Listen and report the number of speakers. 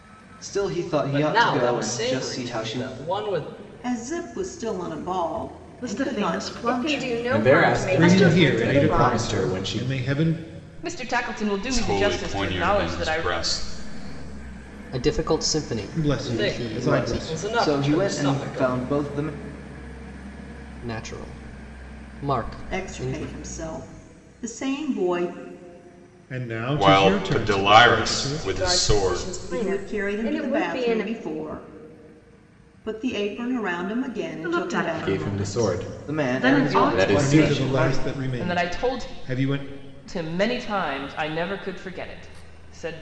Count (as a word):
ten